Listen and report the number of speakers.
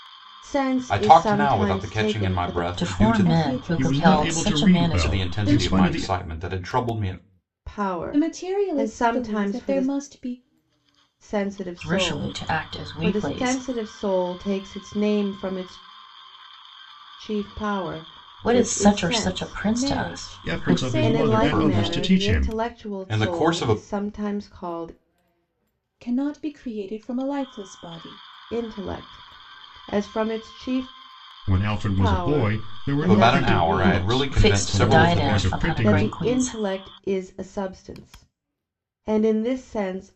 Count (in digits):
5